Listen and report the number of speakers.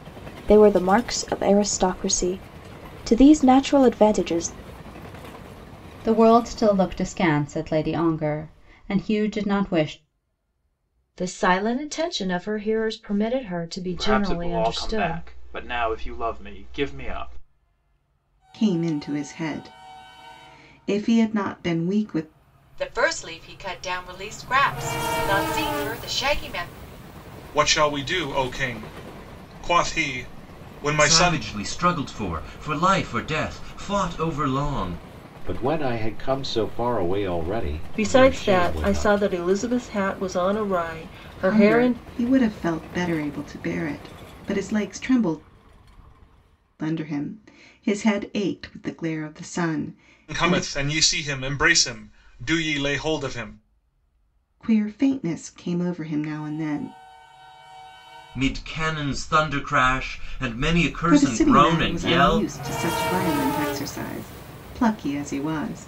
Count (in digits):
10